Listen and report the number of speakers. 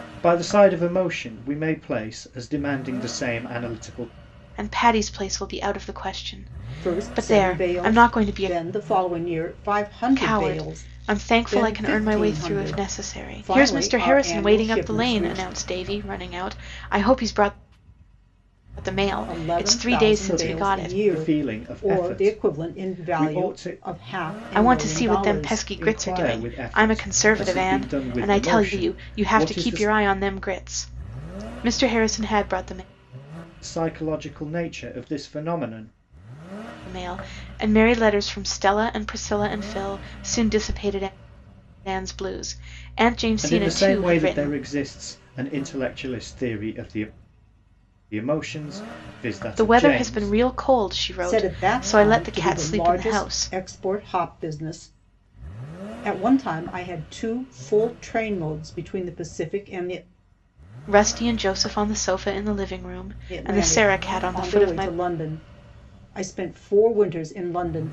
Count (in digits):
3